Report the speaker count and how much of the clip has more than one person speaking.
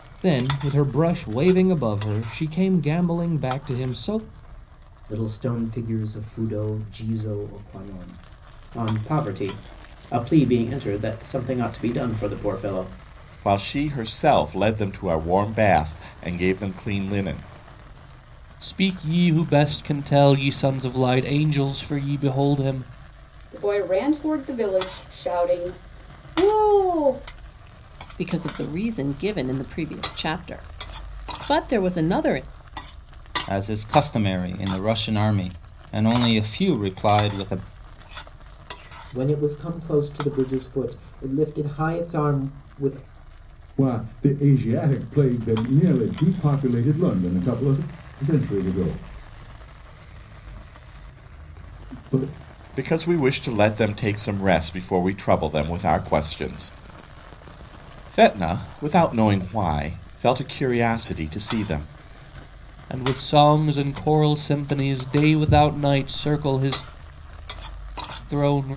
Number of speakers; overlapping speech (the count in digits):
10, no overlap